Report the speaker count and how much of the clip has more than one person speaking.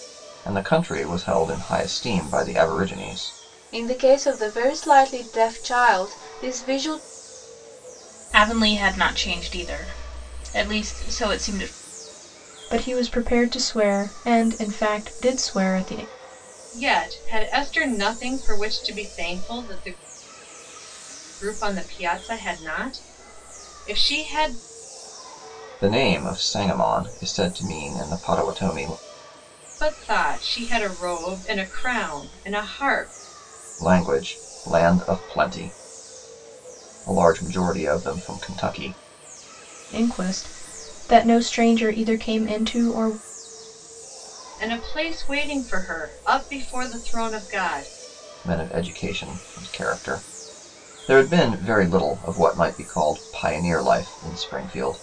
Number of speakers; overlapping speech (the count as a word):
five, no overlap